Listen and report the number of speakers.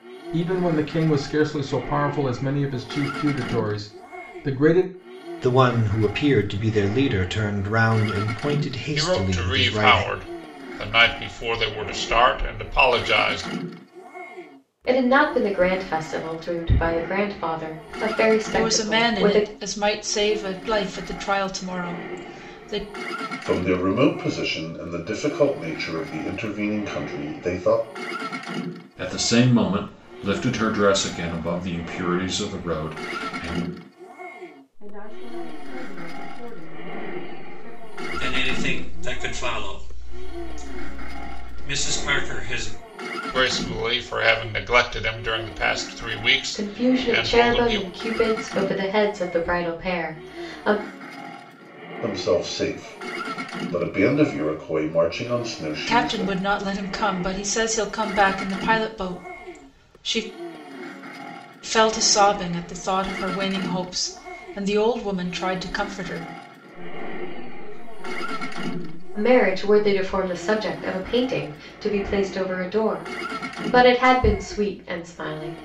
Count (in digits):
9